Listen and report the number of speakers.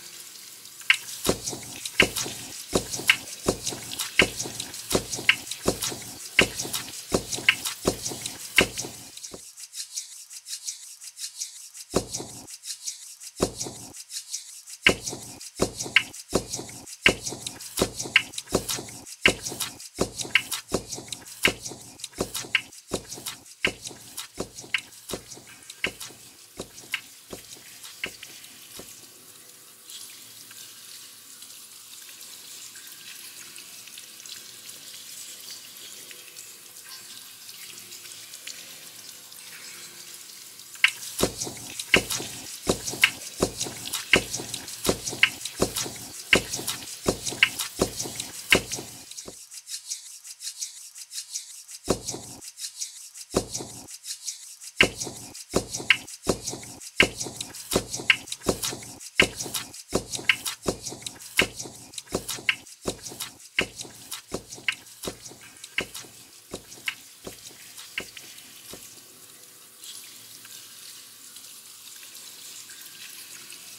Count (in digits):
0